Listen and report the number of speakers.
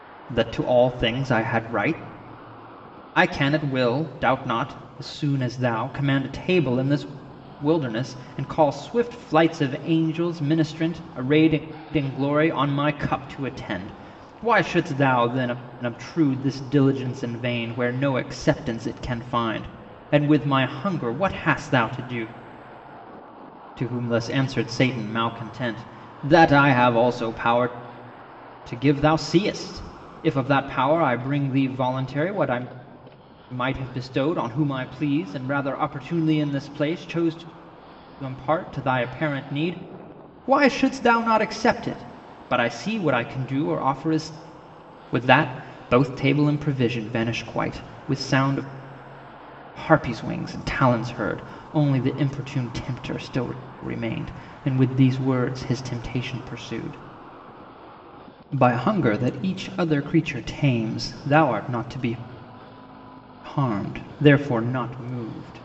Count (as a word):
one